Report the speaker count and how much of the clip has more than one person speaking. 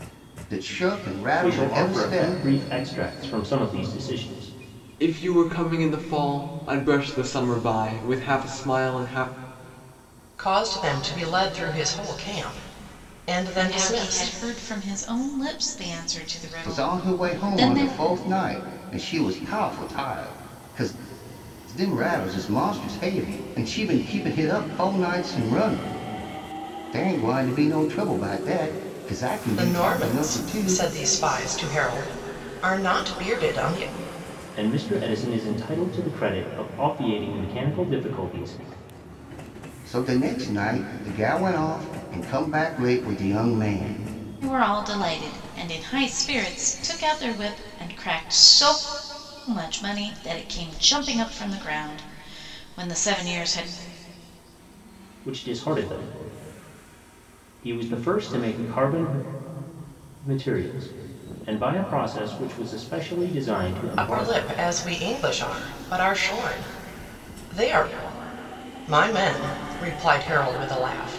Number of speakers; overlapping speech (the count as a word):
five, about 7%